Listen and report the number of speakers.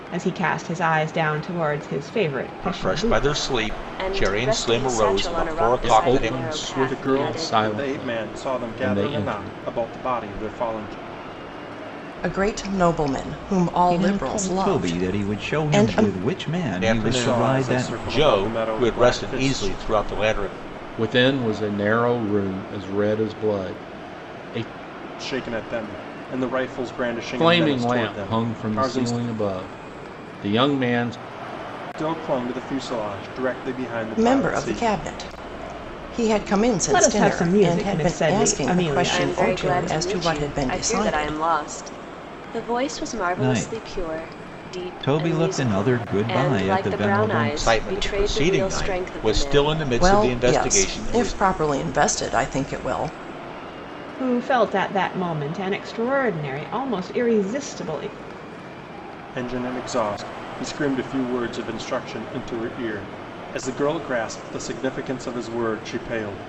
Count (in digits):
7